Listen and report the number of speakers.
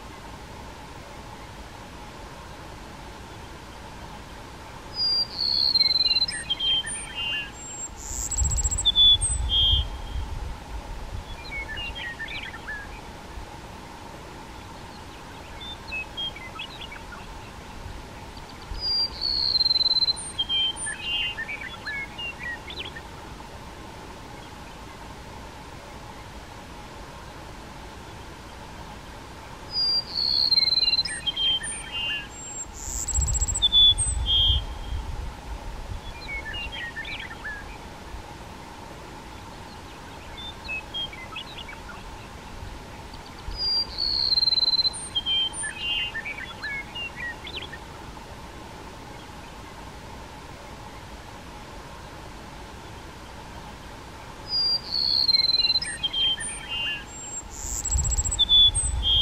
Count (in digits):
0